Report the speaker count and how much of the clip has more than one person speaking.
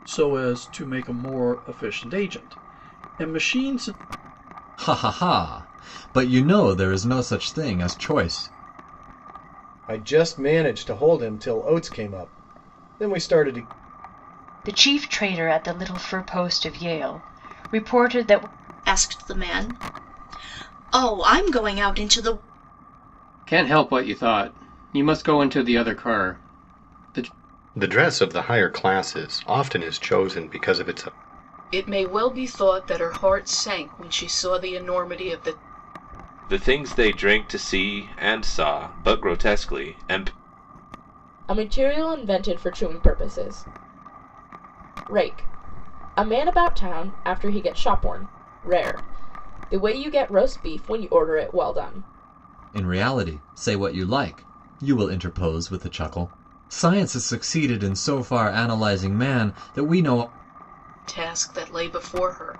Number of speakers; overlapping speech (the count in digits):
10, no overlap